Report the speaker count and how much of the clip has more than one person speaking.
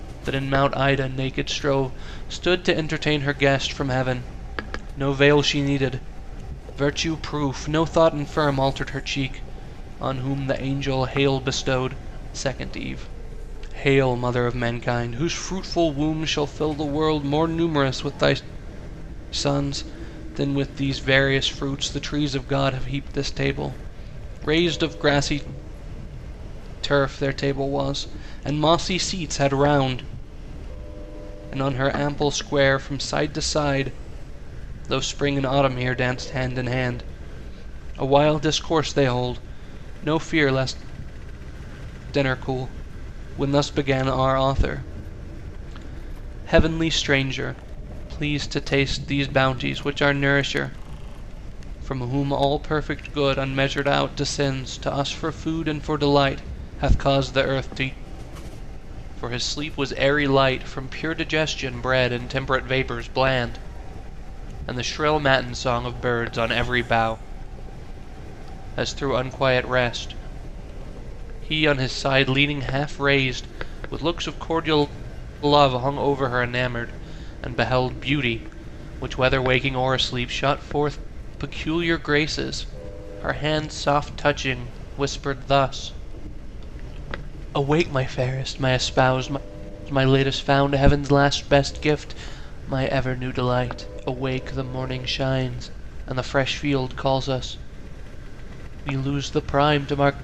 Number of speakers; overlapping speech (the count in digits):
1, no overlap